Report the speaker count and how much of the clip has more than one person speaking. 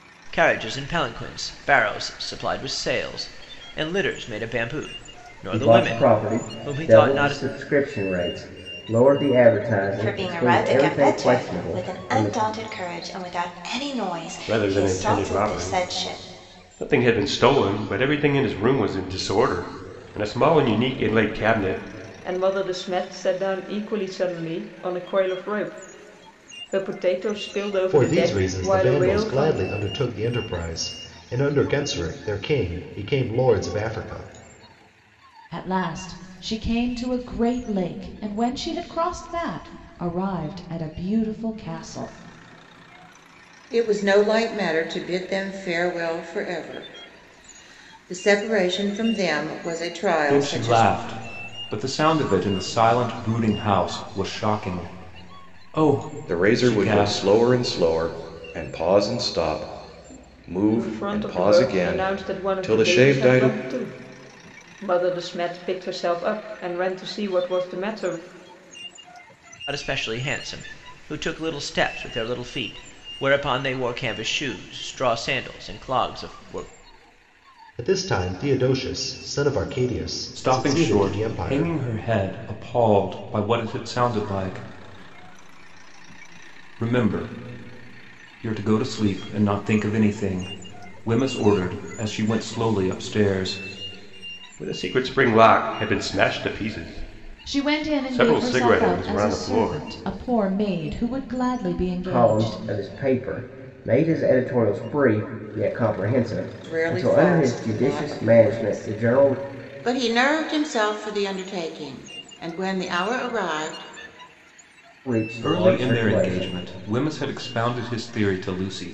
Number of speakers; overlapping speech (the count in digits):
10, about 18%